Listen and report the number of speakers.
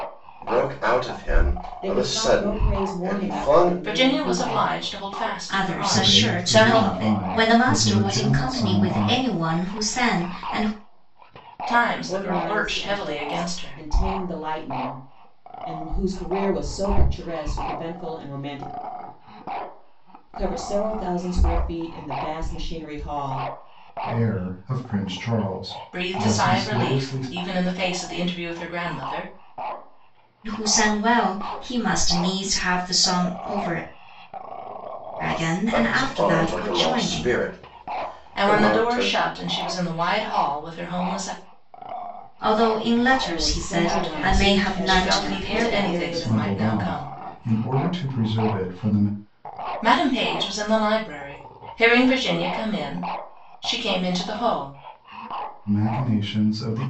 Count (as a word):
five